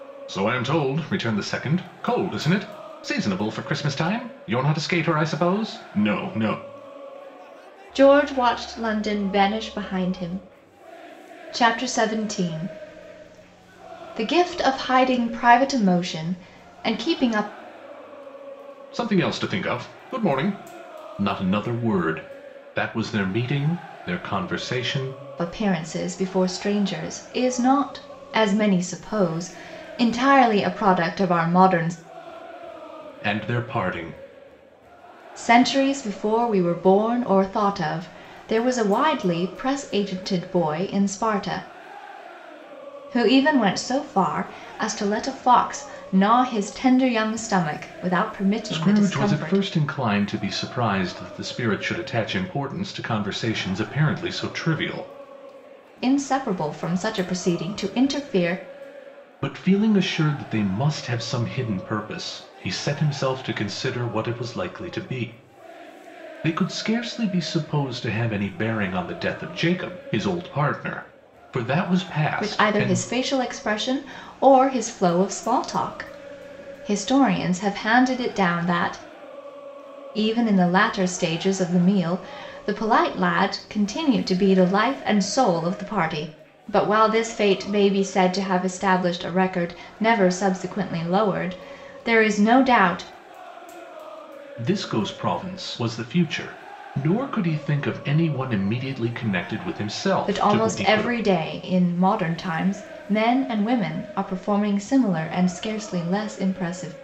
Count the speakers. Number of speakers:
two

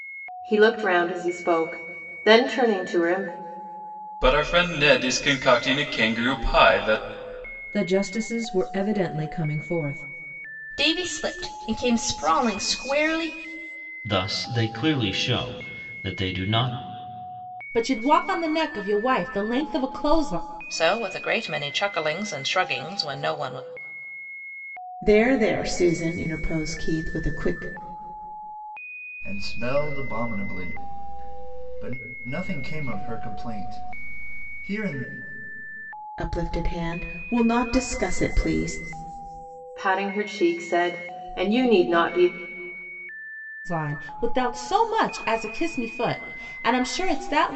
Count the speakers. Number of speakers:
nine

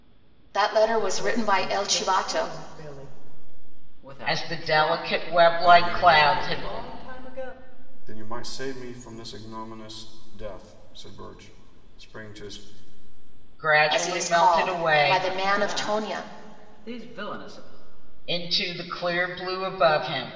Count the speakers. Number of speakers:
five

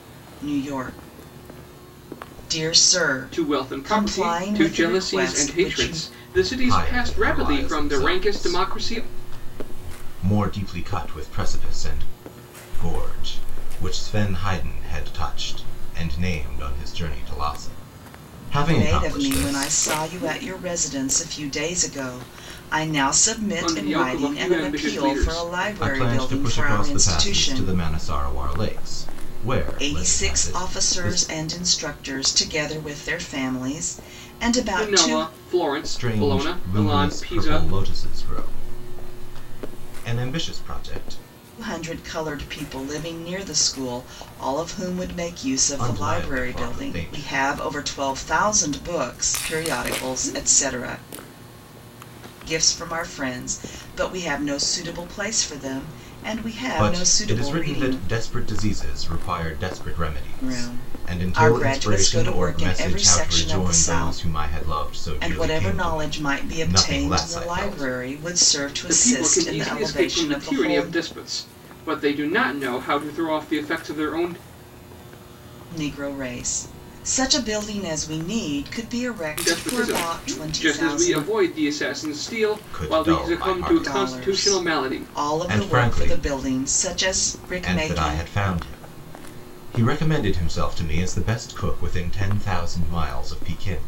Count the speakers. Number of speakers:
three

